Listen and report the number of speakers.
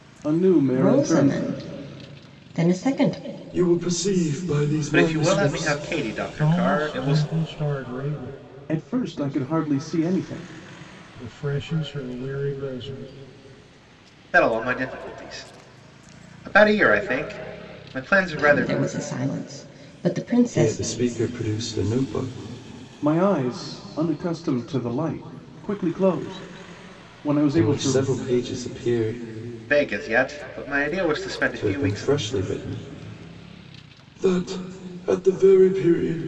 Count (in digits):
5